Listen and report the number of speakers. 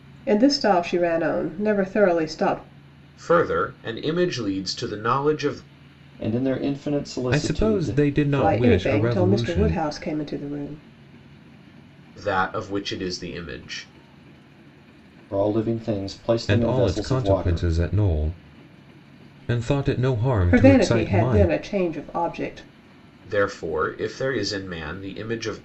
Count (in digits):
4